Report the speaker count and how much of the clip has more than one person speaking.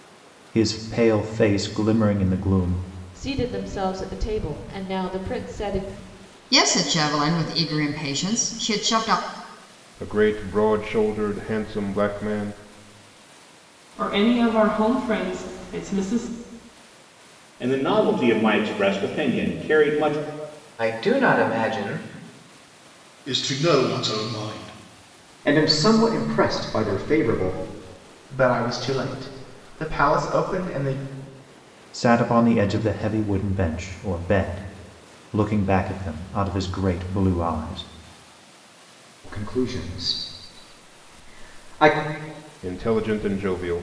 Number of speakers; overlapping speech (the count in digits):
10, no overlap